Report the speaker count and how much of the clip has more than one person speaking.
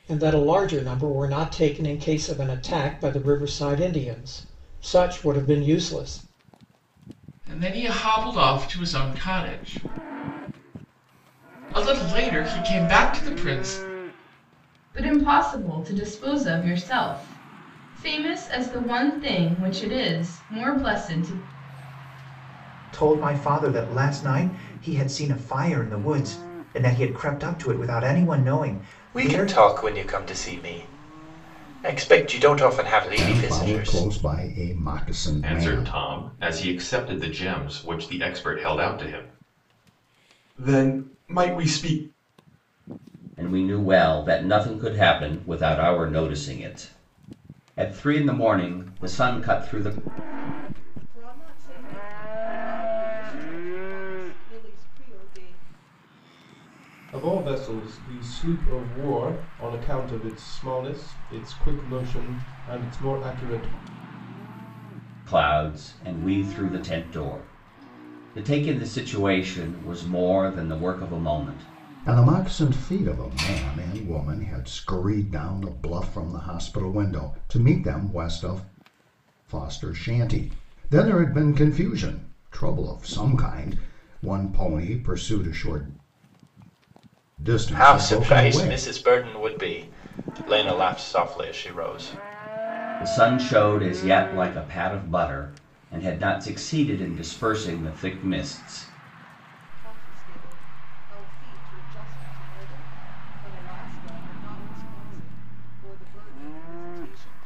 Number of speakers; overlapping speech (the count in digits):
10, about 4%